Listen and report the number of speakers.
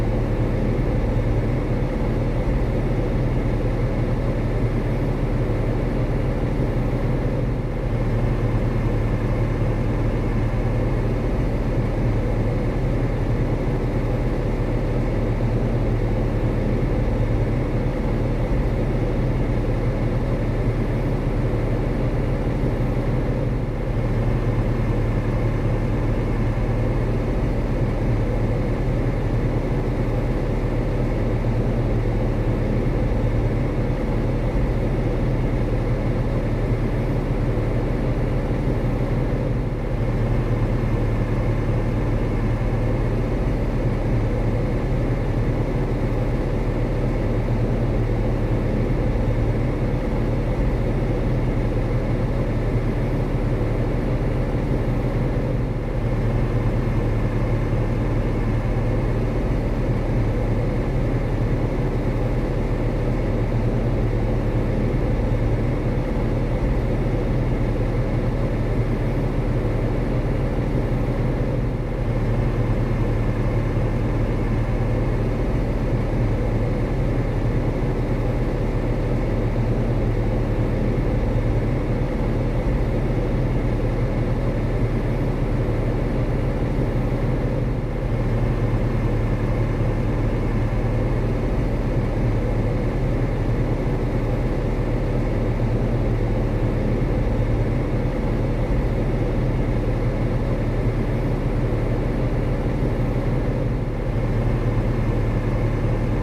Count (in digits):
0